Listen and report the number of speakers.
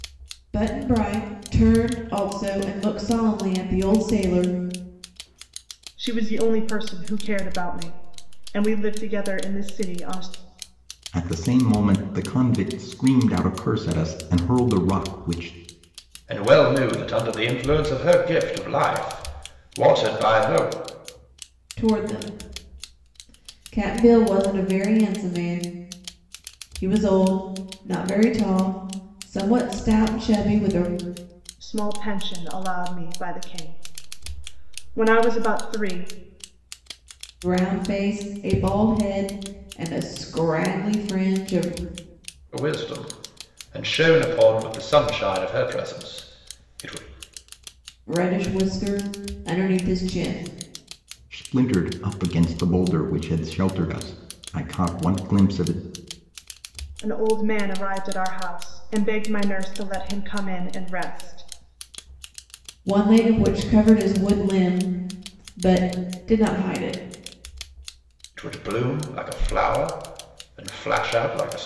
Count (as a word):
four